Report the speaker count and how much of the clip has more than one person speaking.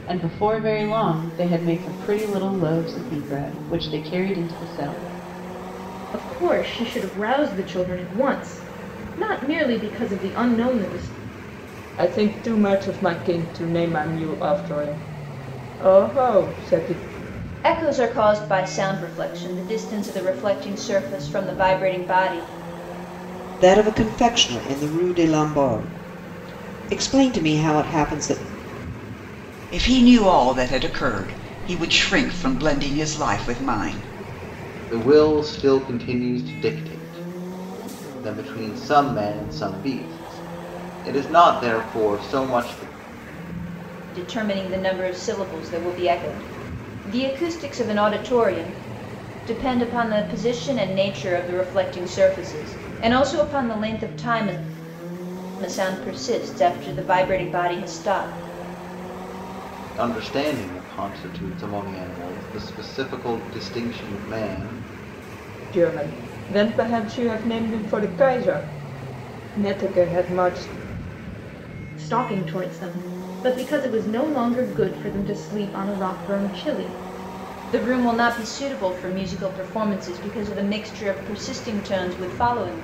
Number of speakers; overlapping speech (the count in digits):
7, no overlap